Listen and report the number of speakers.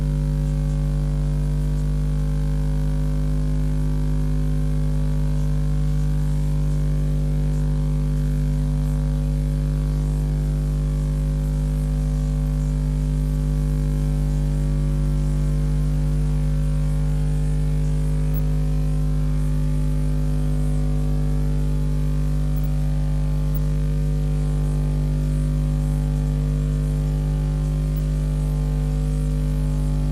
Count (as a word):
zero